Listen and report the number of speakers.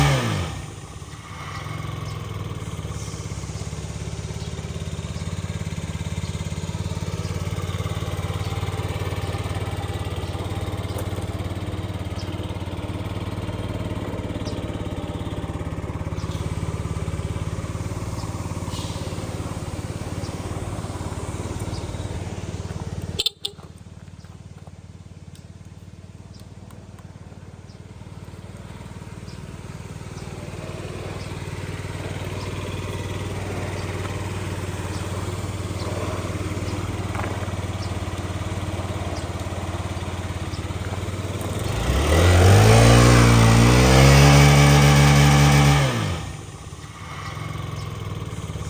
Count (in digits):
0